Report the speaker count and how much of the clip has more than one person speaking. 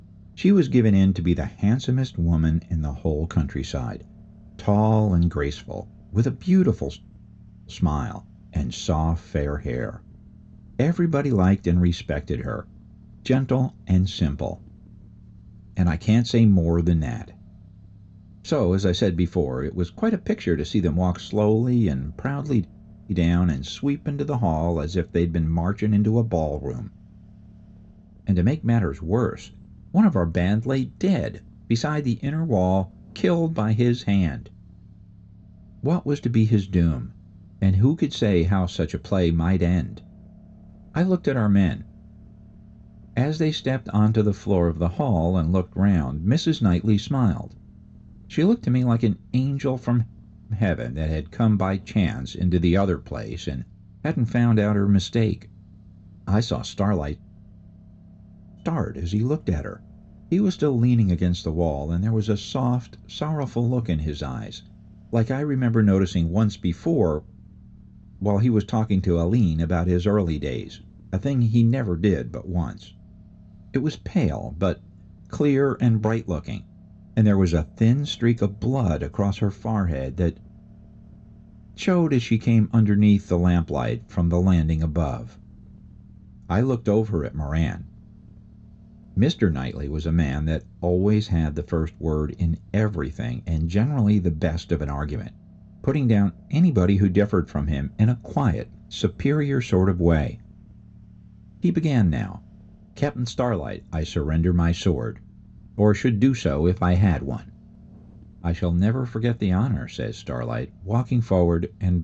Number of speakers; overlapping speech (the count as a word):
one, no overlap